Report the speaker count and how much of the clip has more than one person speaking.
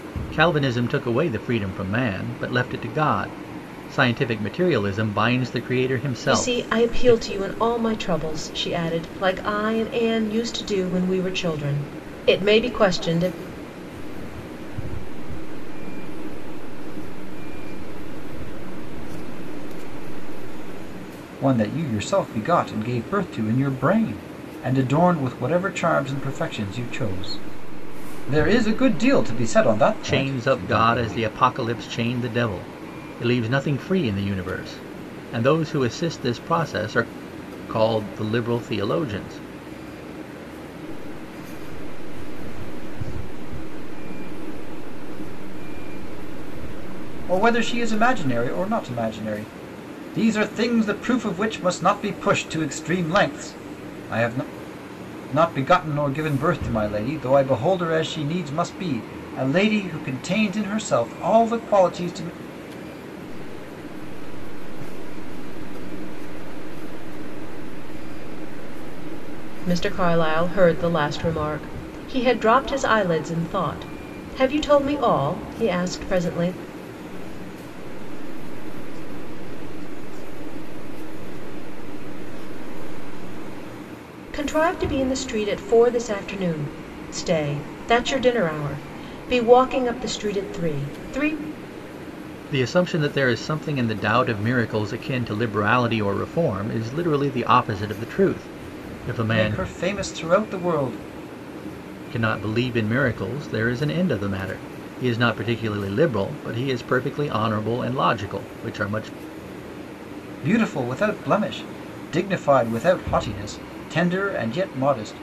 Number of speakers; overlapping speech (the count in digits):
4, about 5%